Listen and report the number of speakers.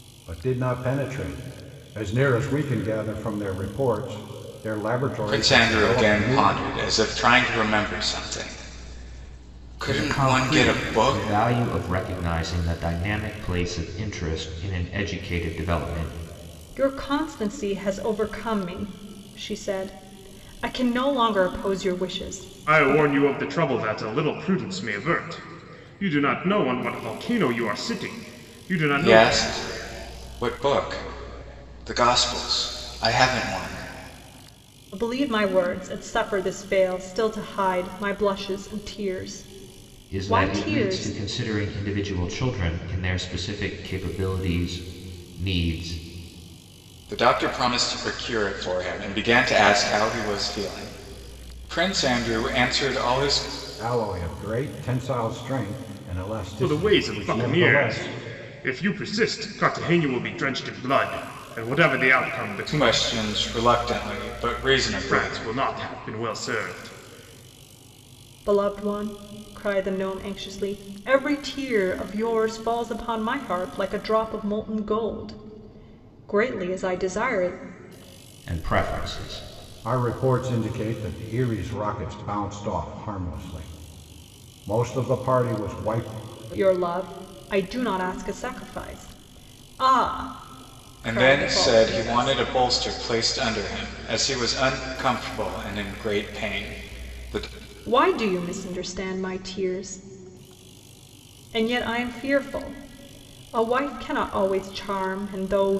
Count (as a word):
five